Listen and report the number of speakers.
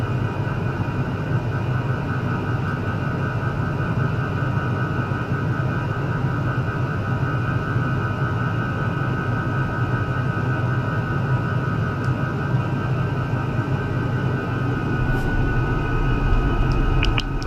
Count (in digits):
0